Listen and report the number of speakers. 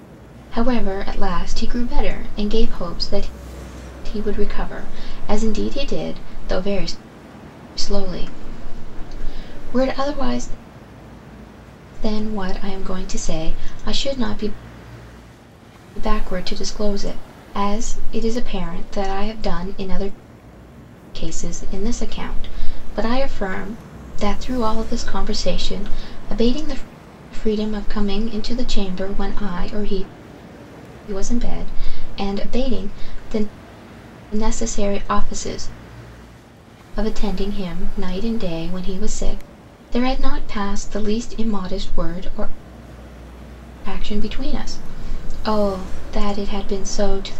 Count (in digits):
1